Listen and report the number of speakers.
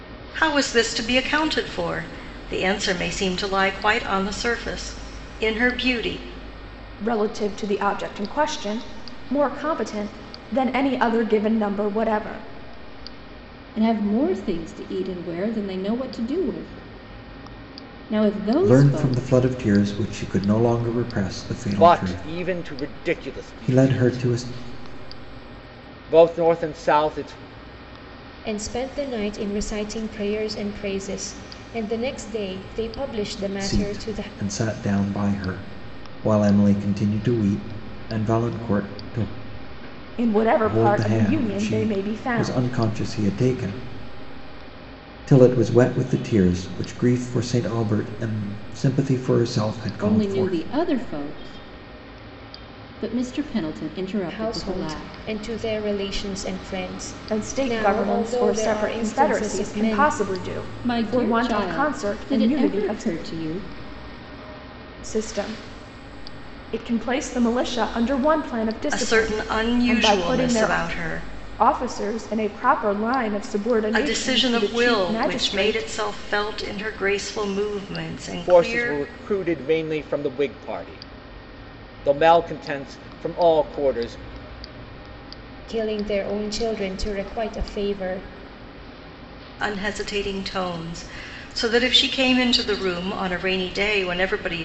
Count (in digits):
6